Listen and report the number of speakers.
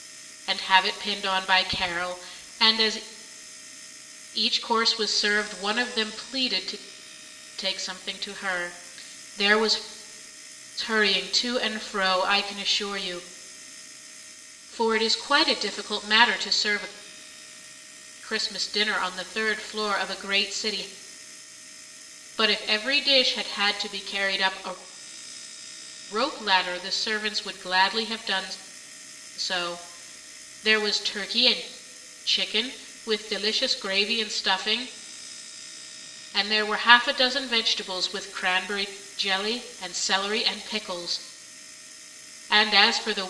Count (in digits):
1